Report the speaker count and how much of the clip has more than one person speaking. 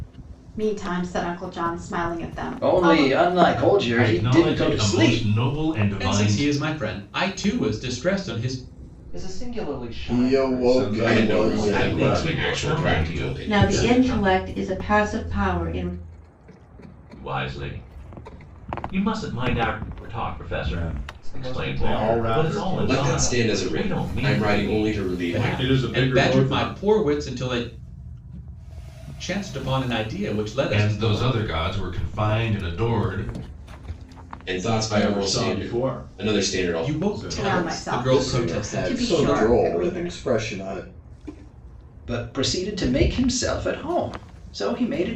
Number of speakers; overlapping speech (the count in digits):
10, about 42%